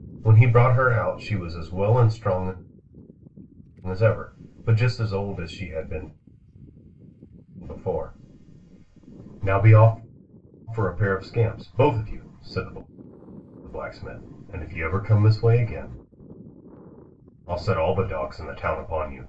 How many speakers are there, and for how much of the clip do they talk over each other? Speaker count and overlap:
1, no overlap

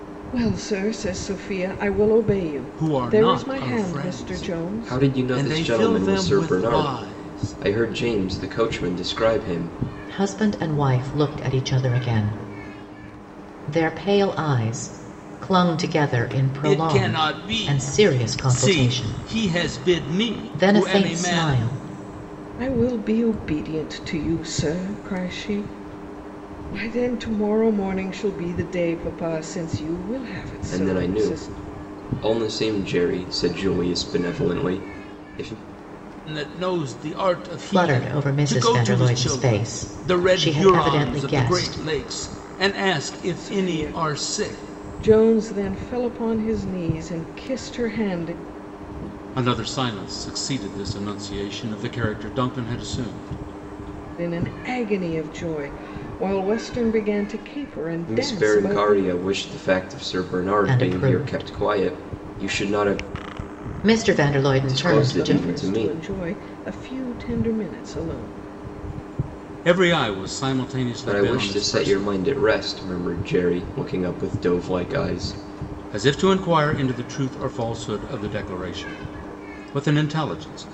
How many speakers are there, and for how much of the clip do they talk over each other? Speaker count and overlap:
4, about 25%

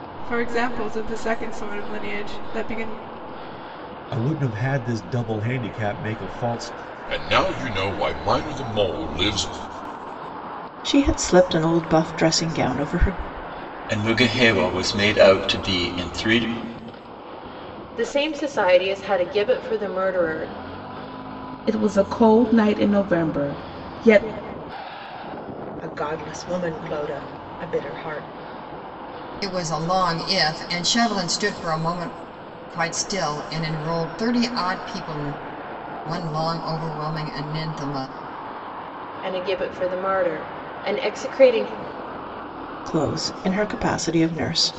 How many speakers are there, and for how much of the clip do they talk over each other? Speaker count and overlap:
9, no overlap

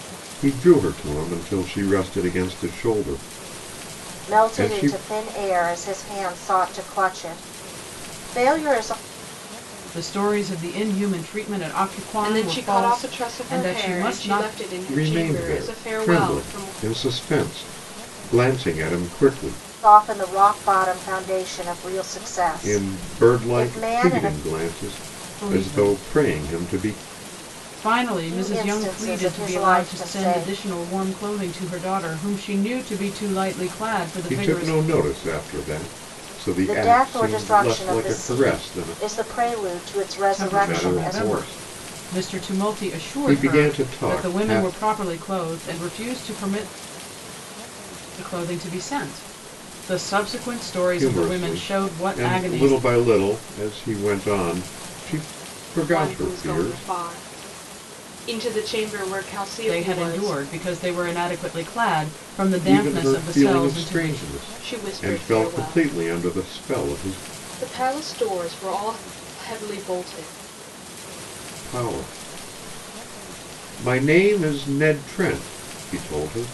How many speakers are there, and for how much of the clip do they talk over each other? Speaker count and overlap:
4, about 33%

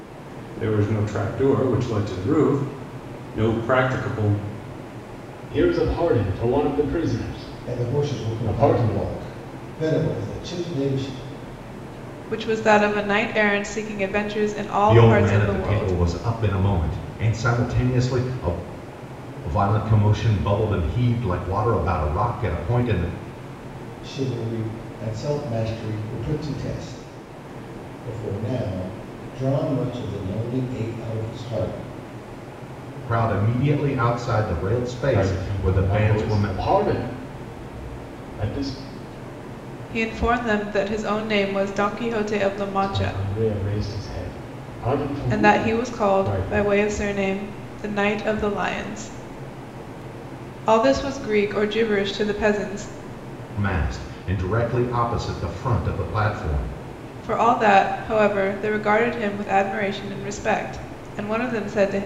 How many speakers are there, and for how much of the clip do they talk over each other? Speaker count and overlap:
5, about 9%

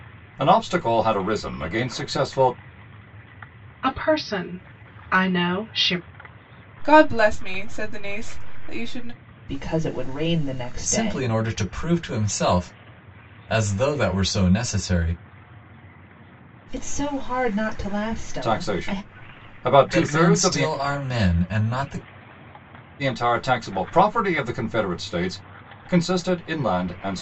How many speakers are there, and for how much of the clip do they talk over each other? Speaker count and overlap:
5, about 7%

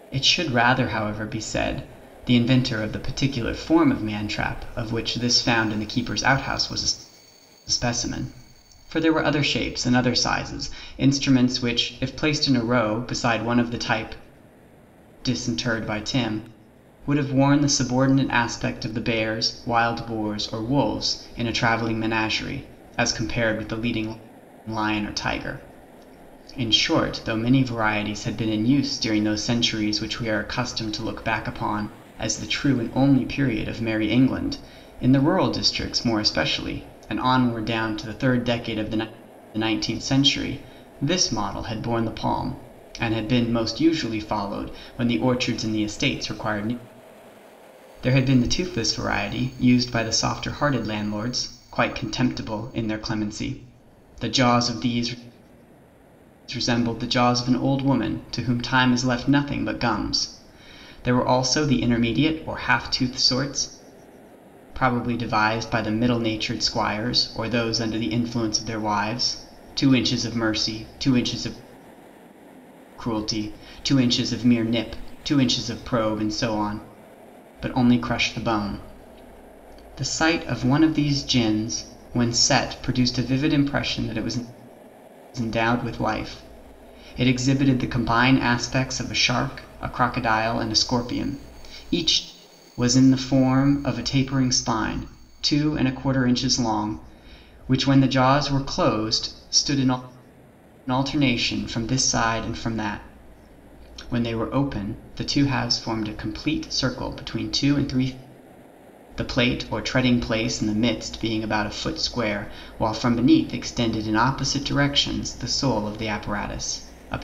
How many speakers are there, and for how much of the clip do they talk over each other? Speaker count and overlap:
1, no overlap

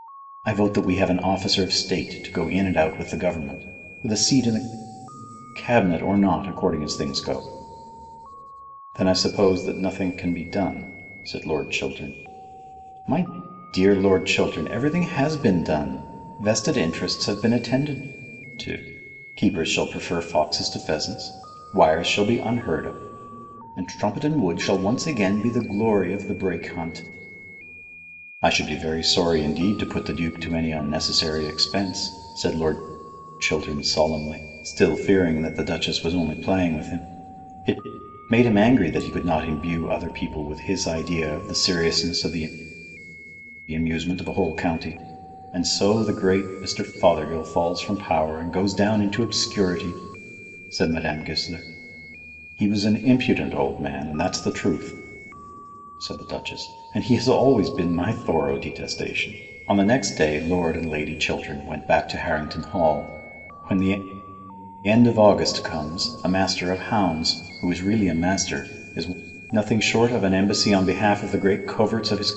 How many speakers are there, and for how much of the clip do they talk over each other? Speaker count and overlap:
1, no overlap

